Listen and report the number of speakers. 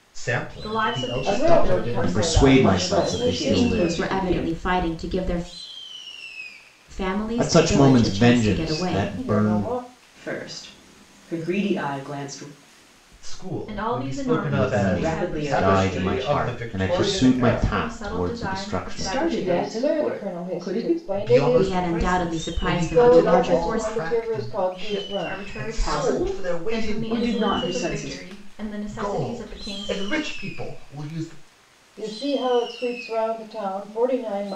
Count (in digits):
6